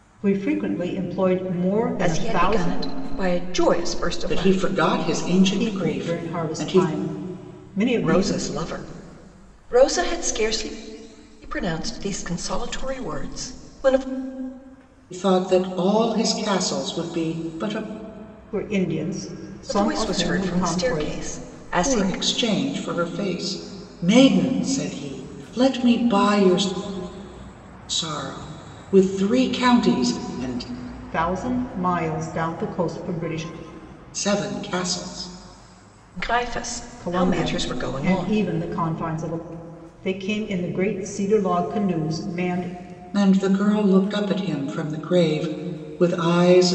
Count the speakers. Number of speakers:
3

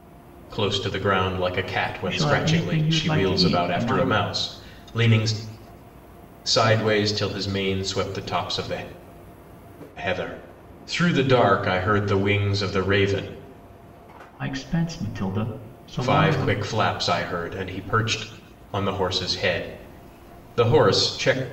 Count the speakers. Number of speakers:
2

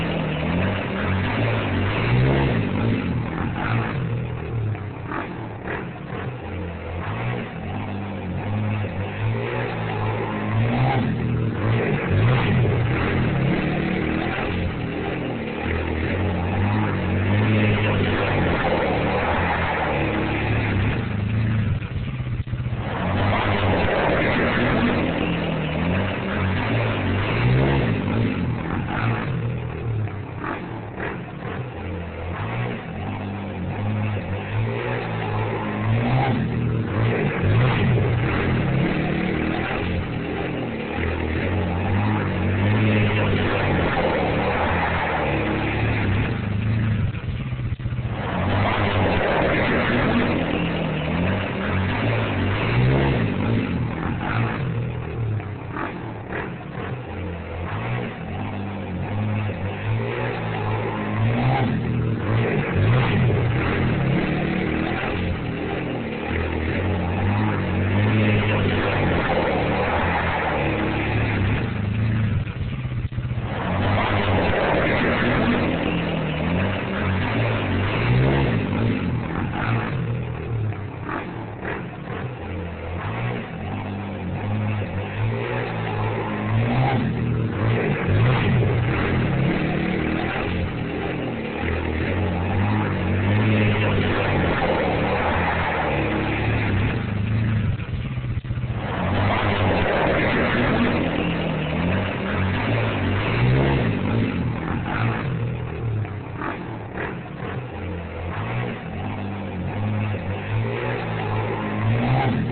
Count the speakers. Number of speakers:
0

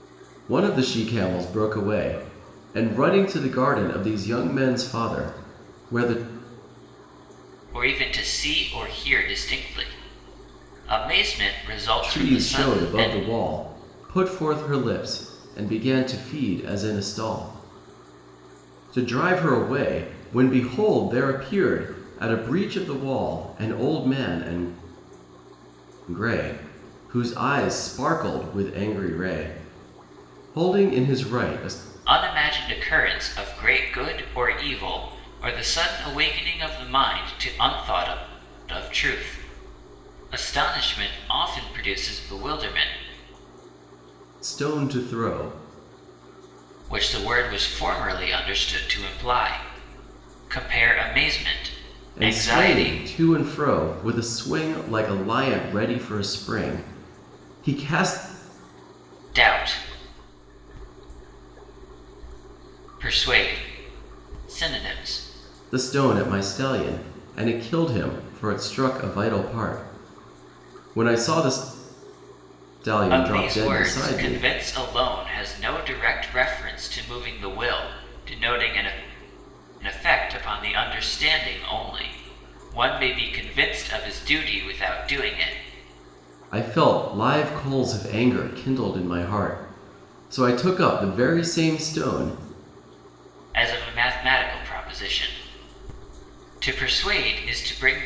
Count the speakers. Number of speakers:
2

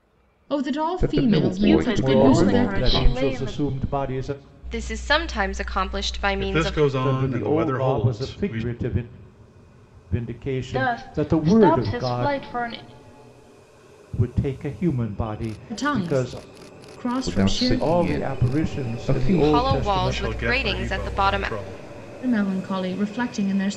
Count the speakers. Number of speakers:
6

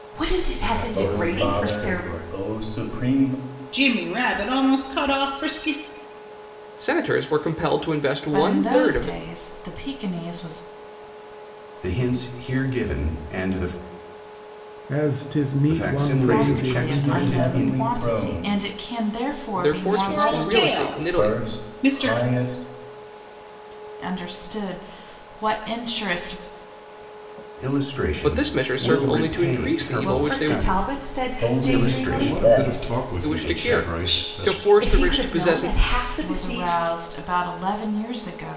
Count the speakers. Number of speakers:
8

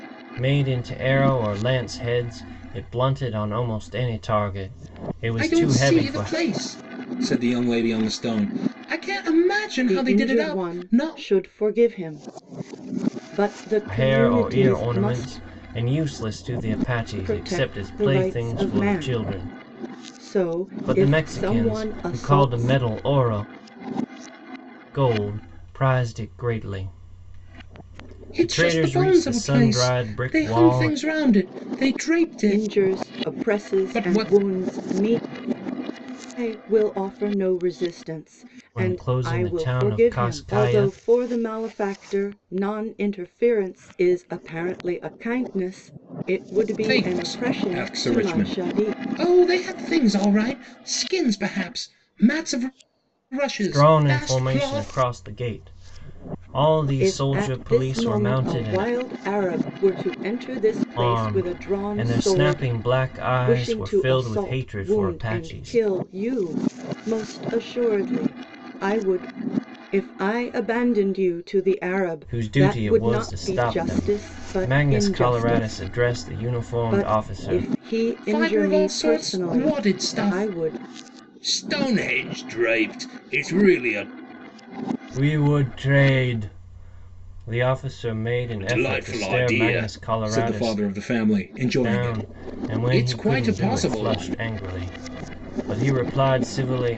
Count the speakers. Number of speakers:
3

